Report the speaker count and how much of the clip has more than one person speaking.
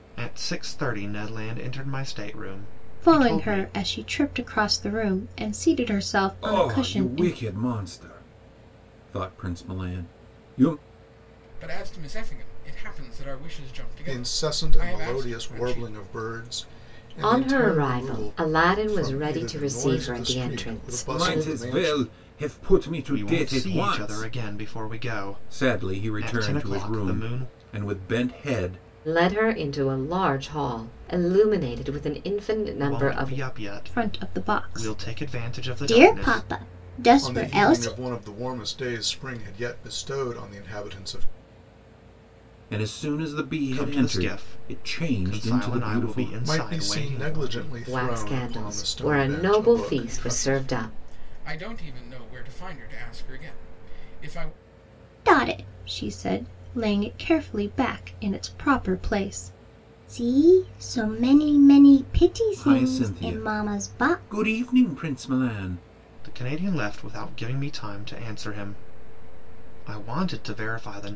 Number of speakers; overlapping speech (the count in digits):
6, about 34%